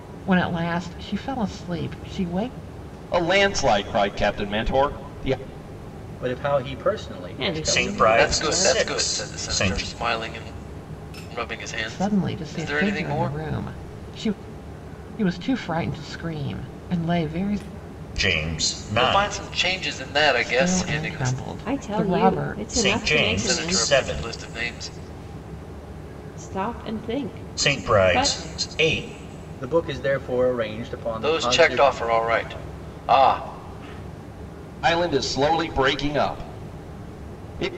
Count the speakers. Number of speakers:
6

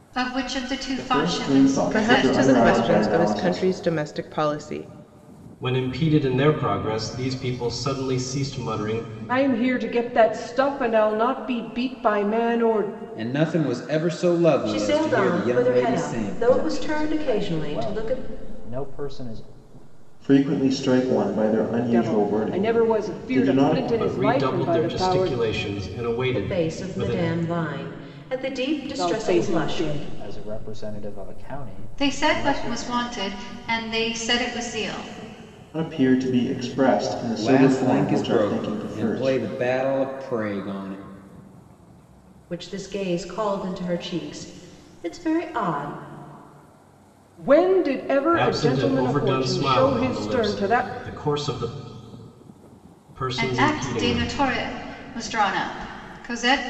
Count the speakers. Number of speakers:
8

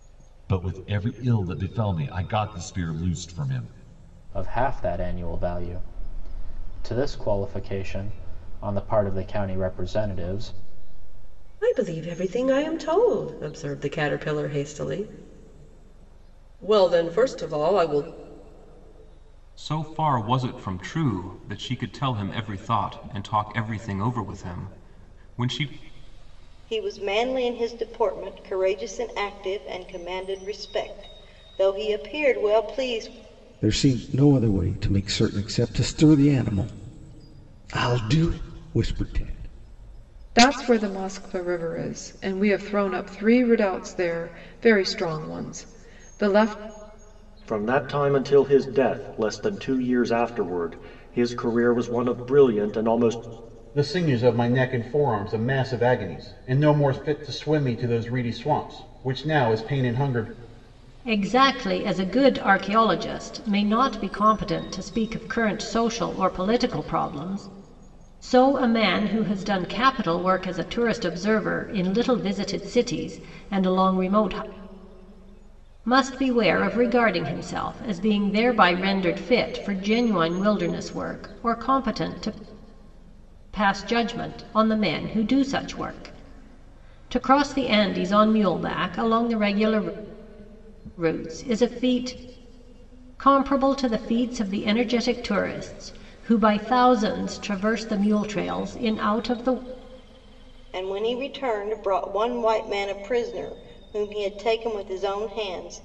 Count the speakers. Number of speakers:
10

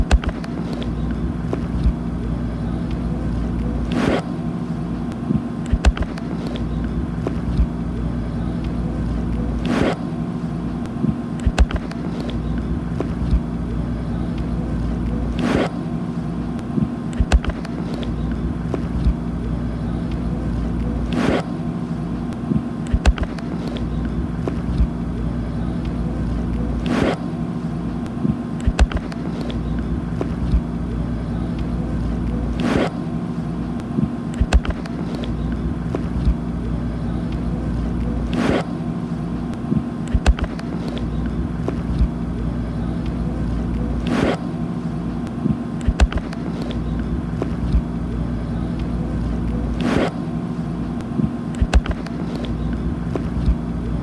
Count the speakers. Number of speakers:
0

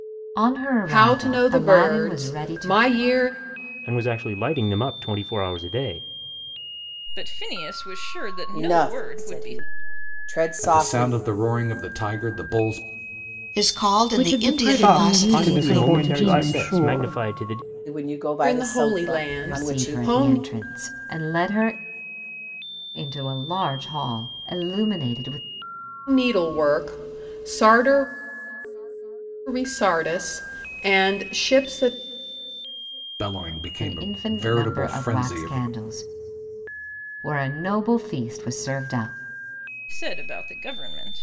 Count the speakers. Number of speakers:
9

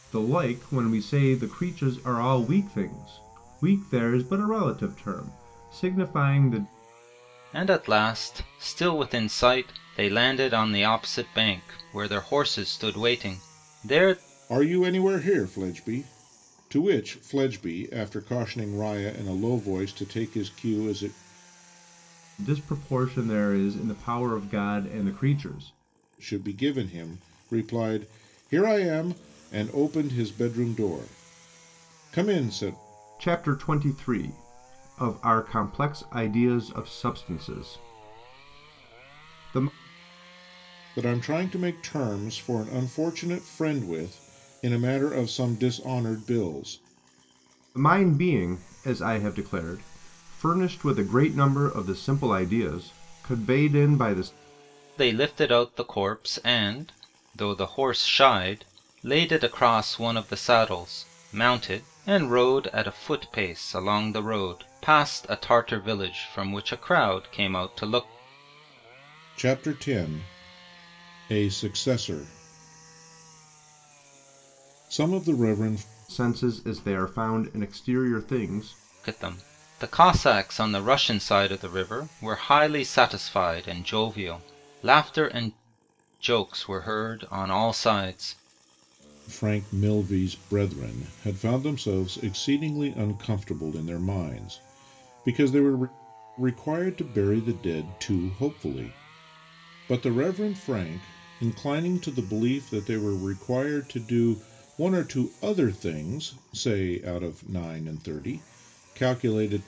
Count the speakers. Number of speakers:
3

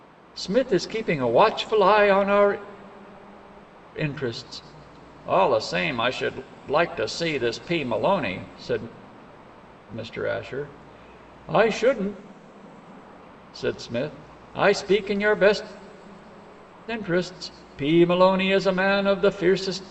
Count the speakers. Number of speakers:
1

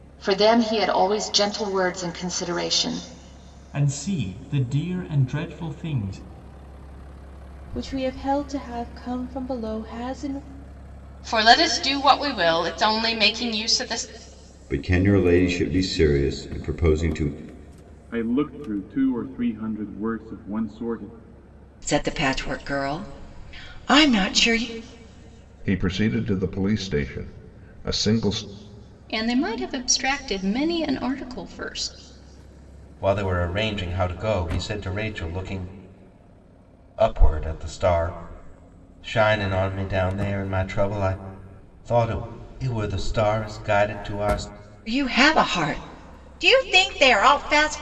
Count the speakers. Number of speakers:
10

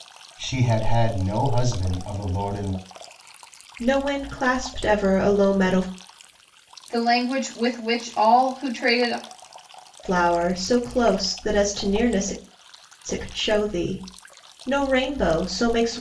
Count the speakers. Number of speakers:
3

